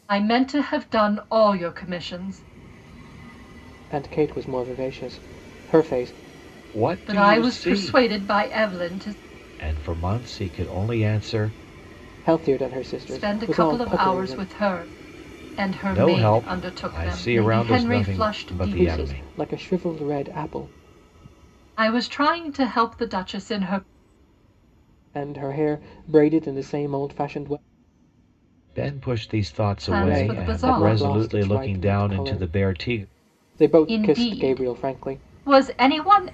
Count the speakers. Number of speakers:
three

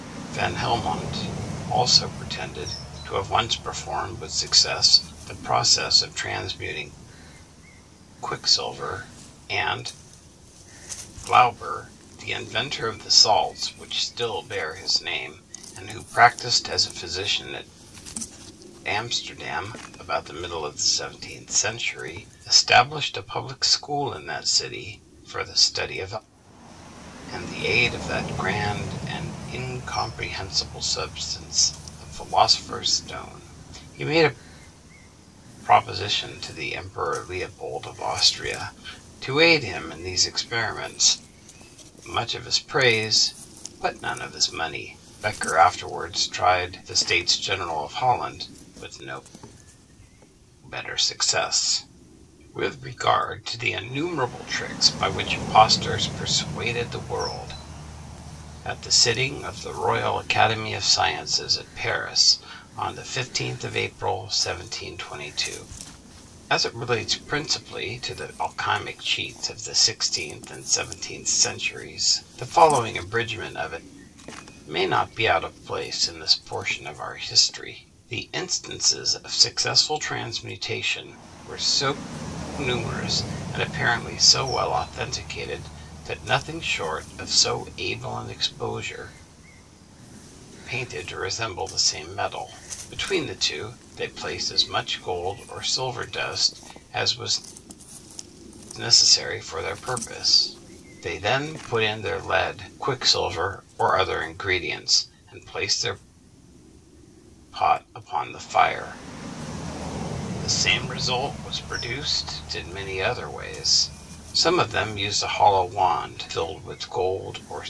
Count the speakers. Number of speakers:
one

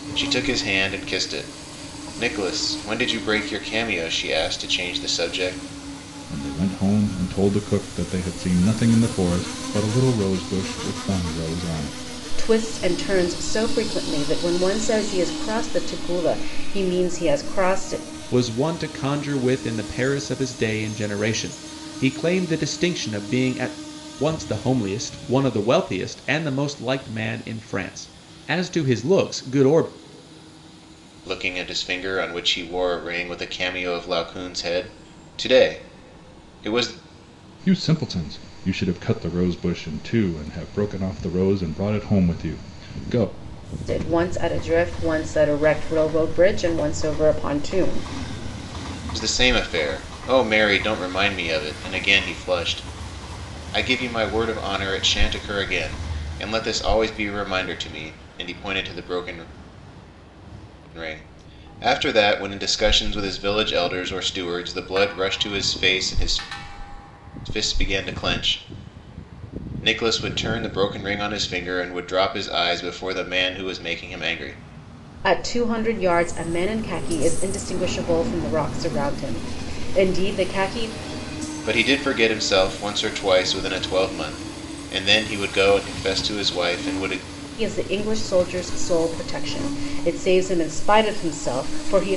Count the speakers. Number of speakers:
four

